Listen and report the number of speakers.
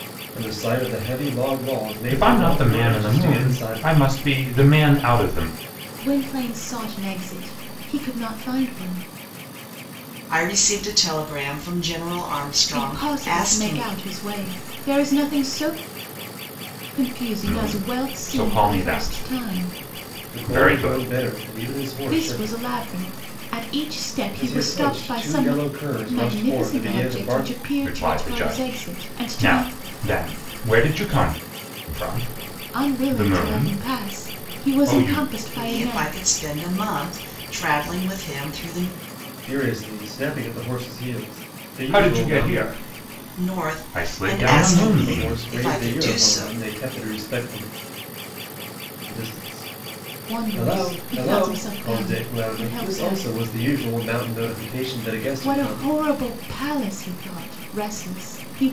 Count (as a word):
four